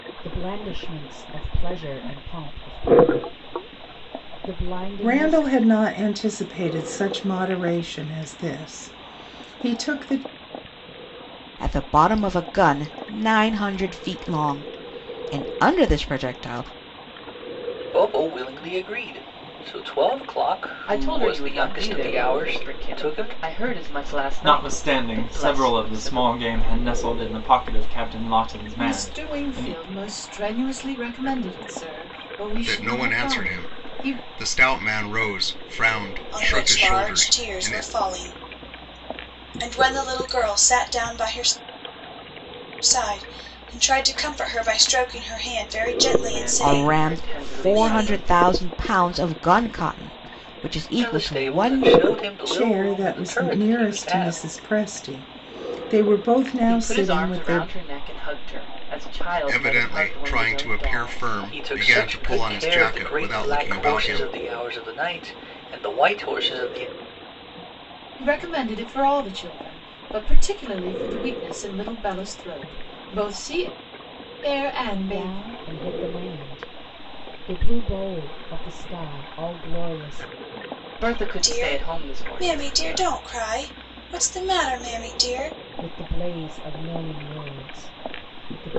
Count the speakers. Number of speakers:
nine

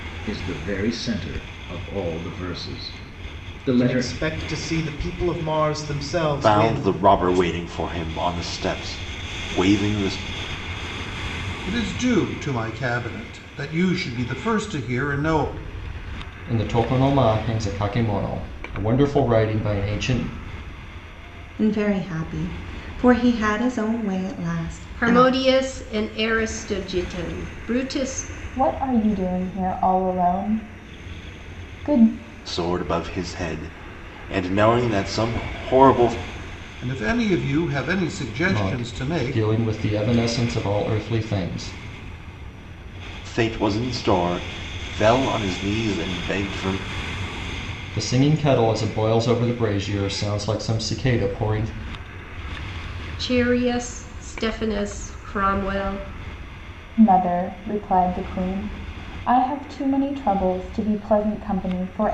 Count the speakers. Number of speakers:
eight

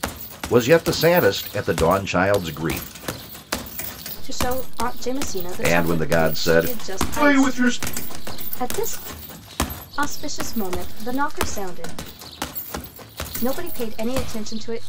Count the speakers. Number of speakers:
two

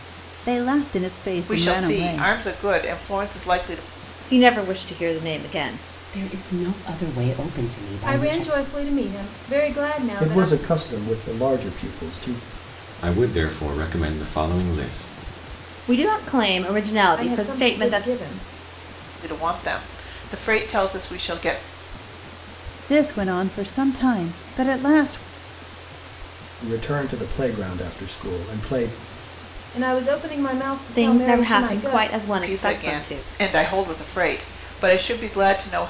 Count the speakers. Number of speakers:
seven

